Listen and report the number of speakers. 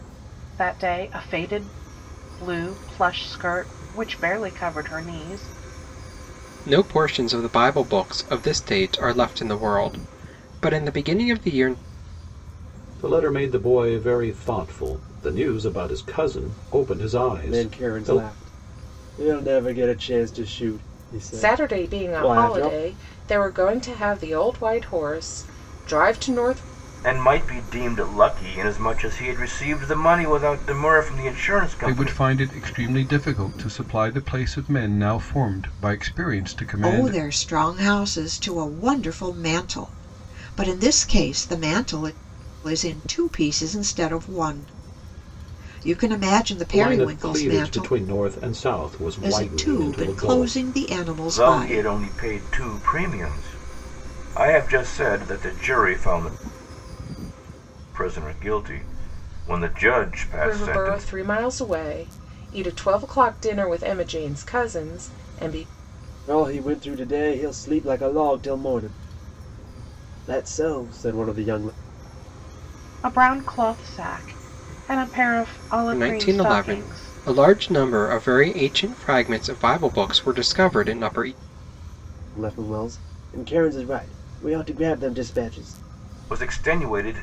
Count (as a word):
eight